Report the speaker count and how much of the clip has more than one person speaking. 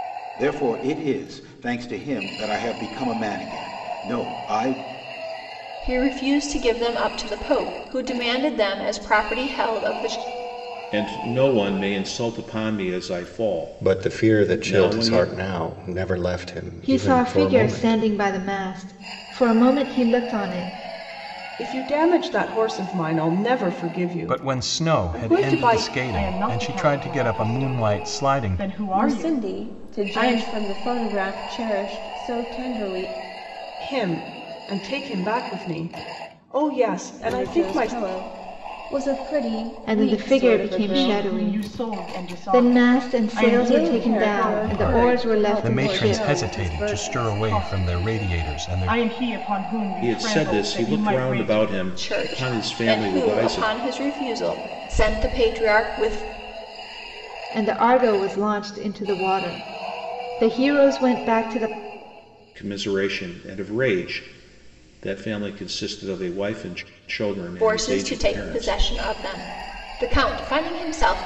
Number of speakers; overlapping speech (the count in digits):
9, about 31%